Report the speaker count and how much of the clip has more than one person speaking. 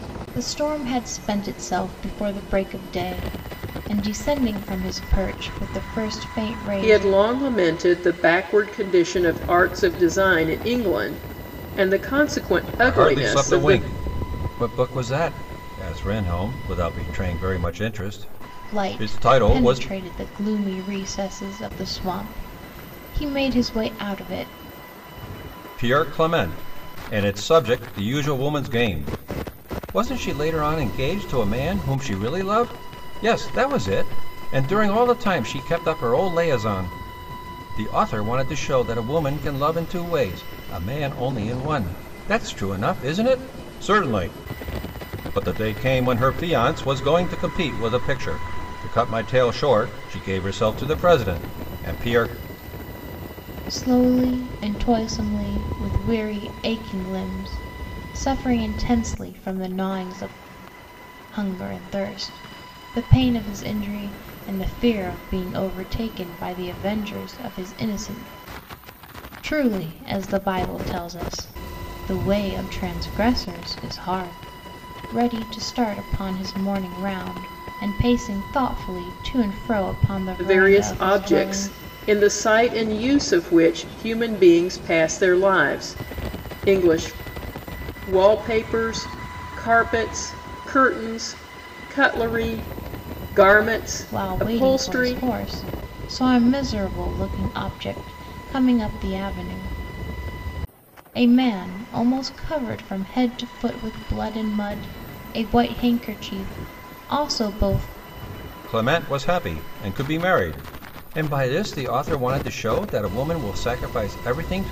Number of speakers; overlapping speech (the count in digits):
3, about 4%